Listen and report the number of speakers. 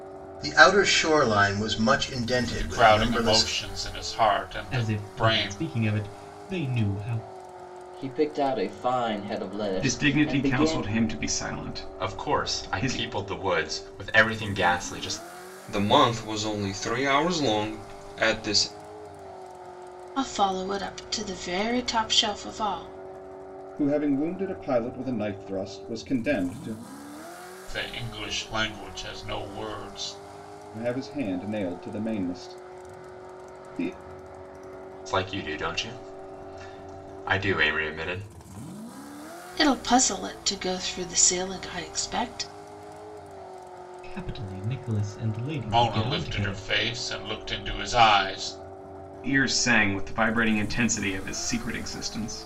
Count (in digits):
9